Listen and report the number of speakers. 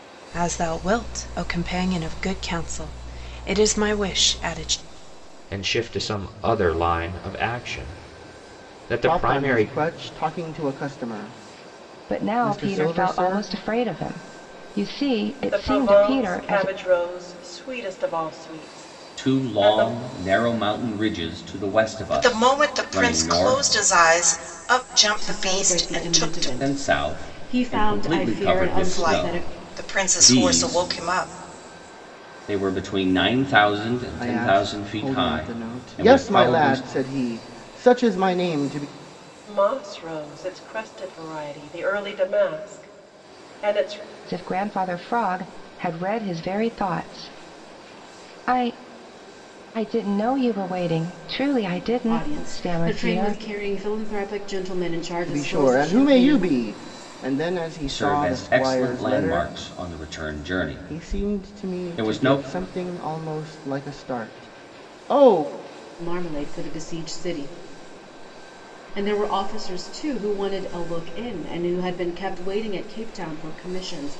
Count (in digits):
8